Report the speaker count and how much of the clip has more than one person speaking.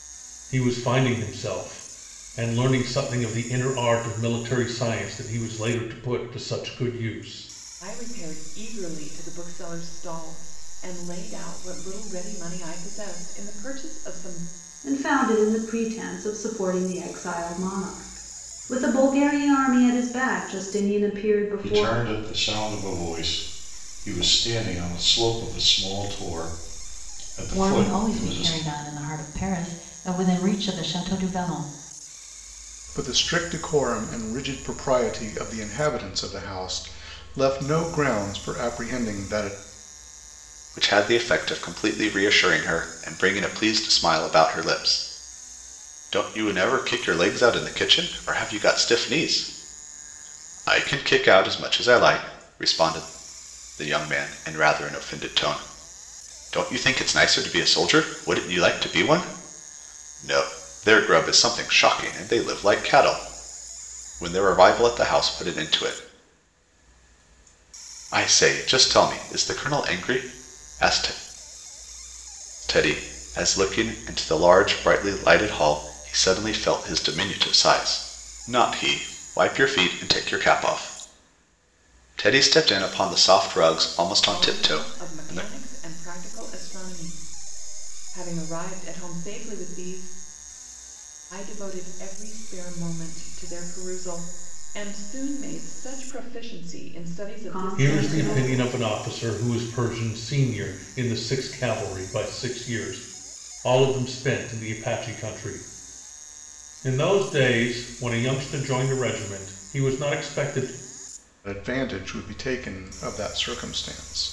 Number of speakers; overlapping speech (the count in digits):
7, about 4%